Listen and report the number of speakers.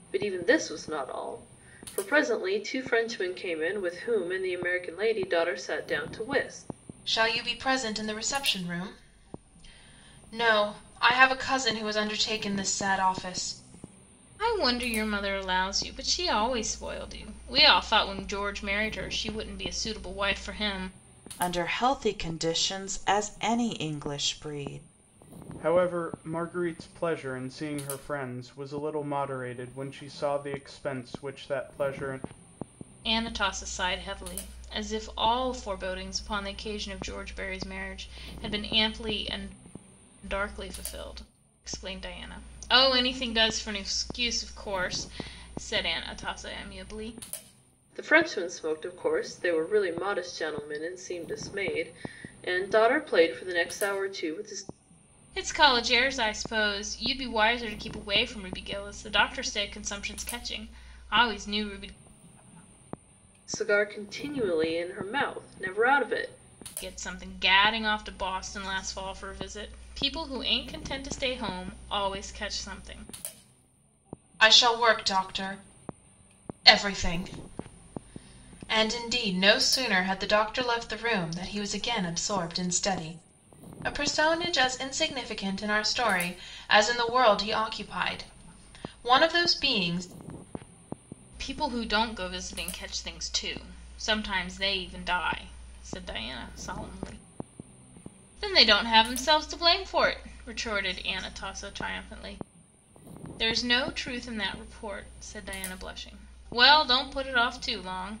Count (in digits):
5